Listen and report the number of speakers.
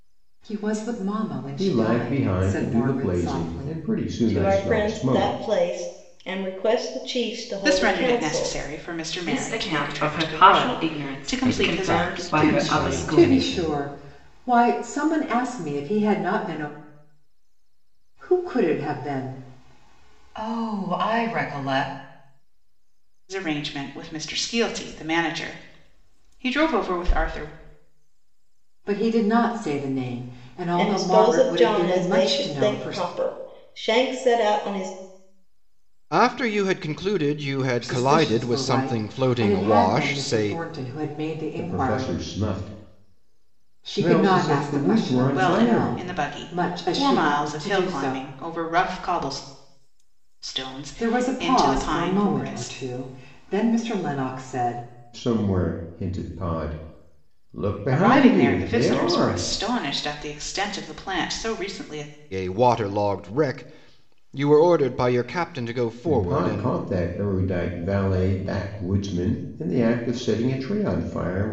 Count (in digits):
6